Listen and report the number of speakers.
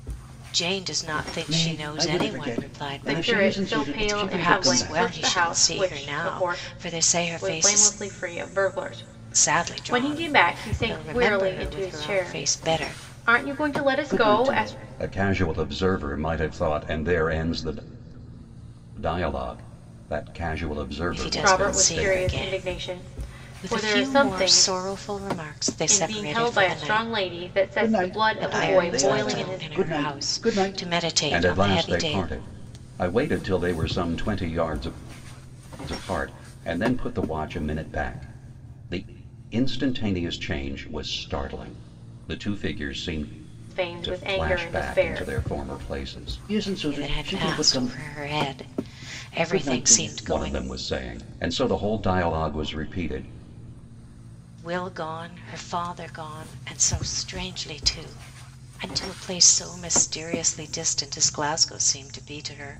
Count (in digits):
3